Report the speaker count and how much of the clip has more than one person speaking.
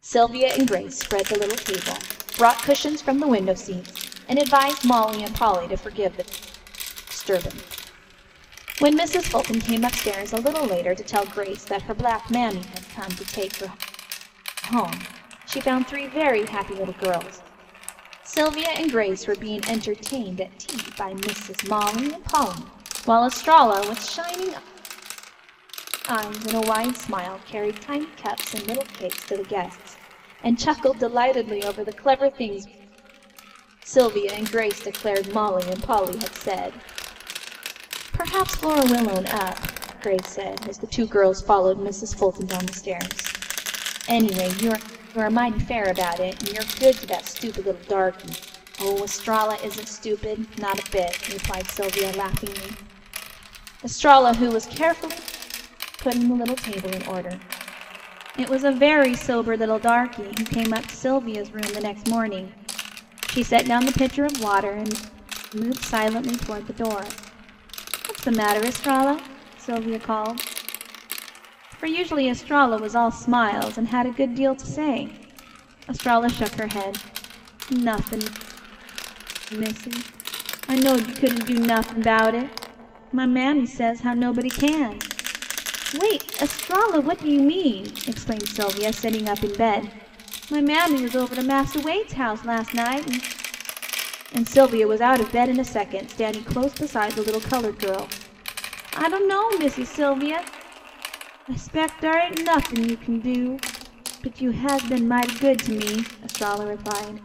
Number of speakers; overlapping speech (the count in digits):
1, no overlap